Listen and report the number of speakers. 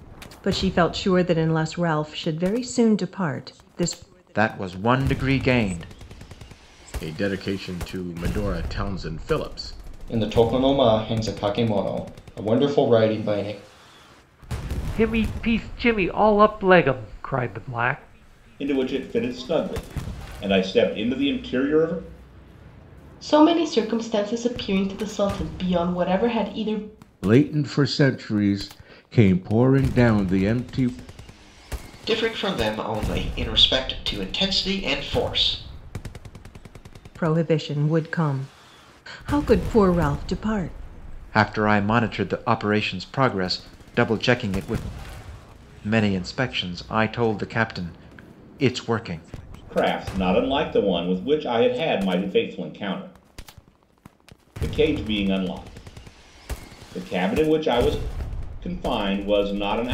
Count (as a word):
nine